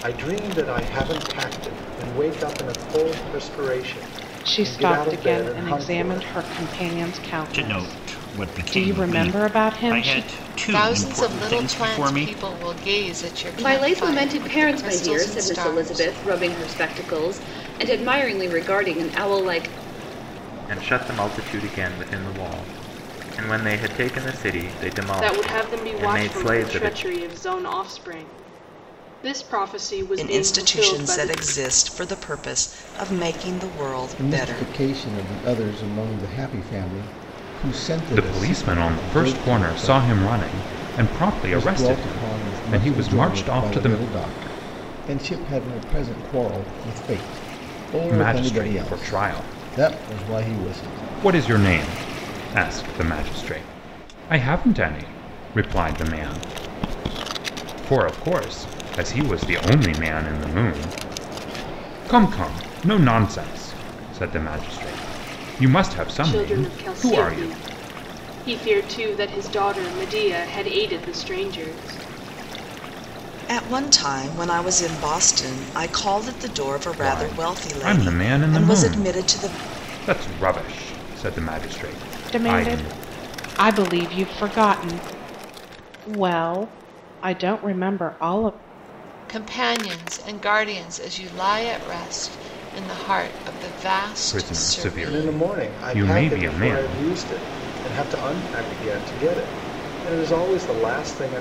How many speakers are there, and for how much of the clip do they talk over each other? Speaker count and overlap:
ten, about 27%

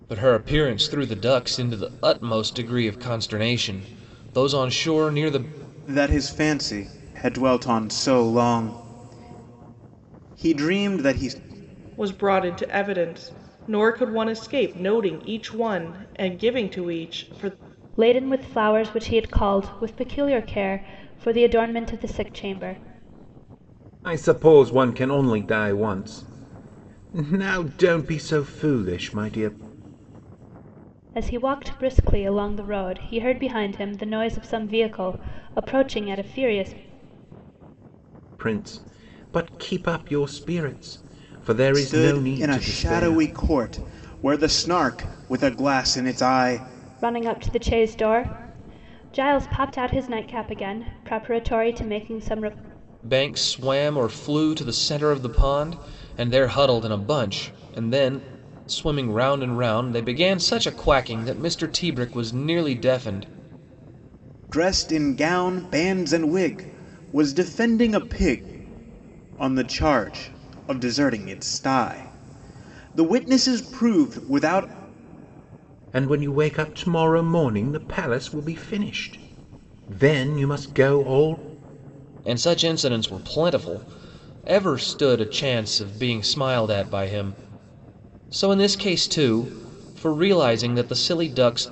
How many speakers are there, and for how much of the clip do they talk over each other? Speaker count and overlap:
five, about 2%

